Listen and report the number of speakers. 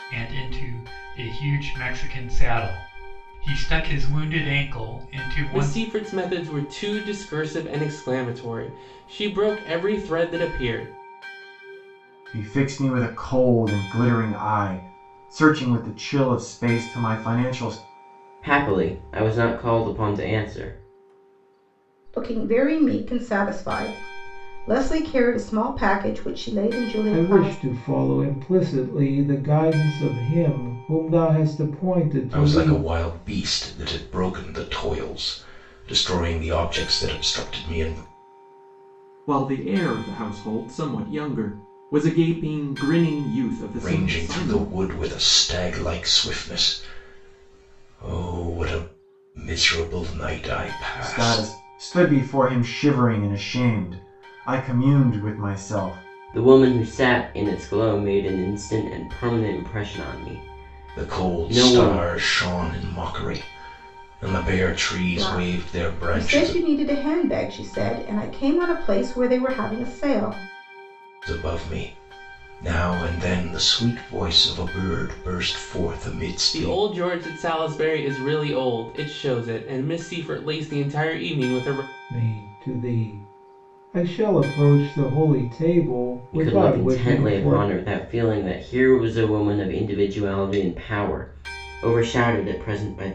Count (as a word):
eight